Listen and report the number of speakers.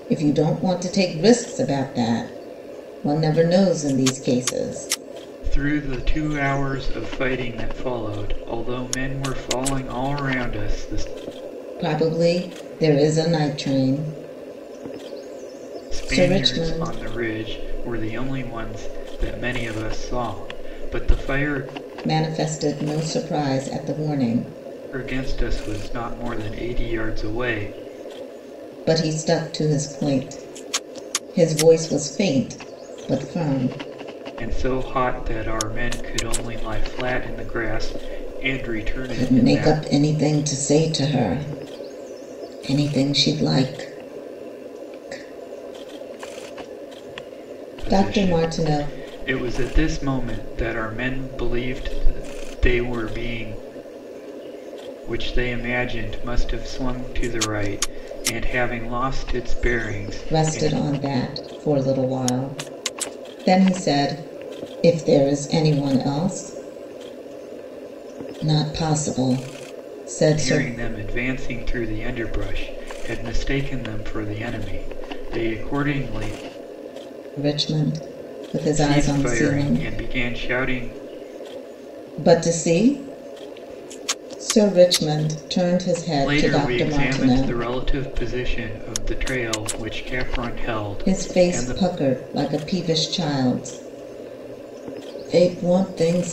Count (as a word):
two